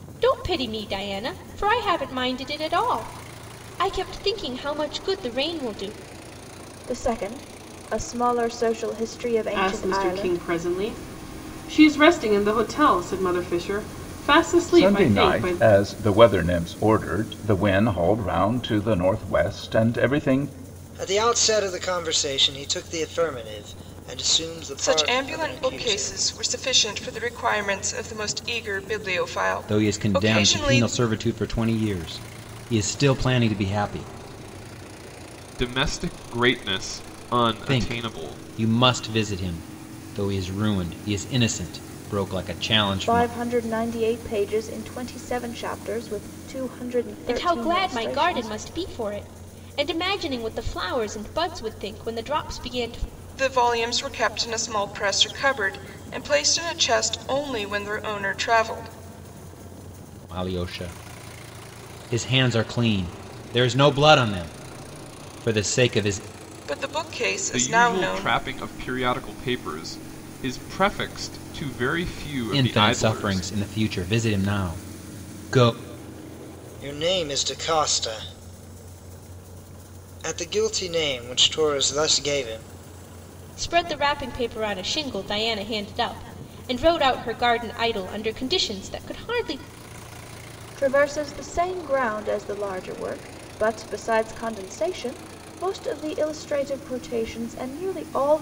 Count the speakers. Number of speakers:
eight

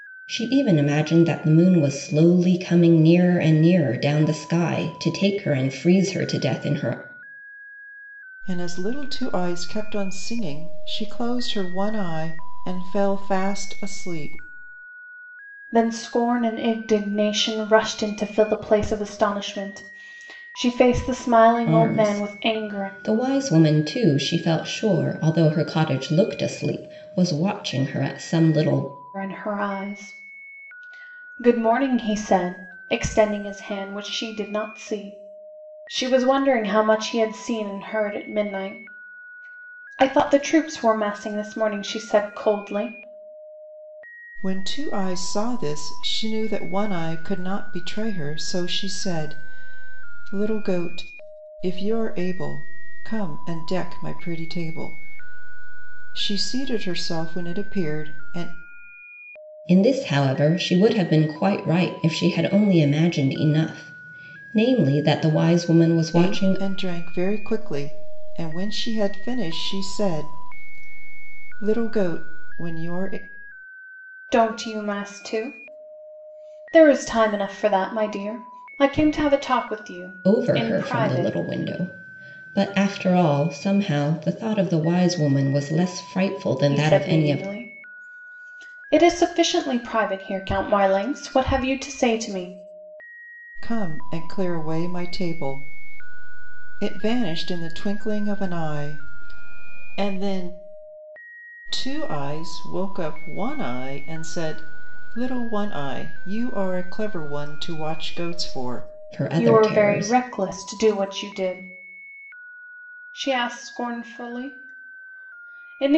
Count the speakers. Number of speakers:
three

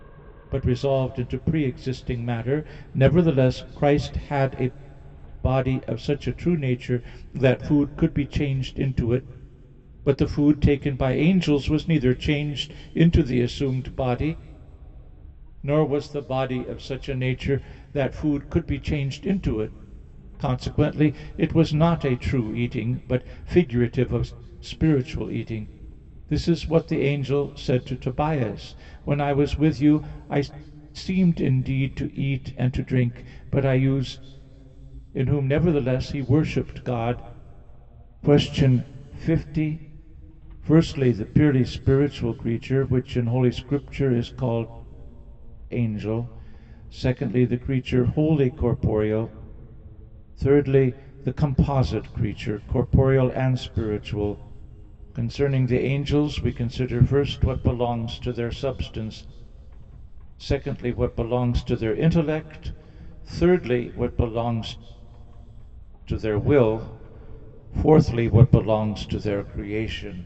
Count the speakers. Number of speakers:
one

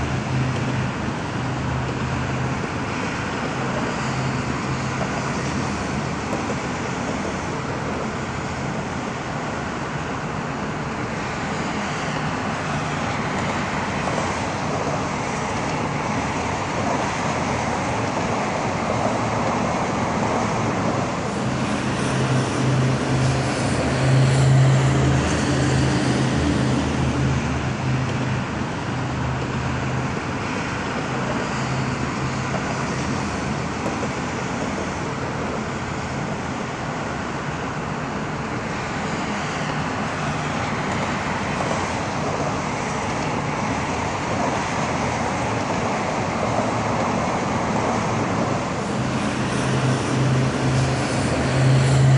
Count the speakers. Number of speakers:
zero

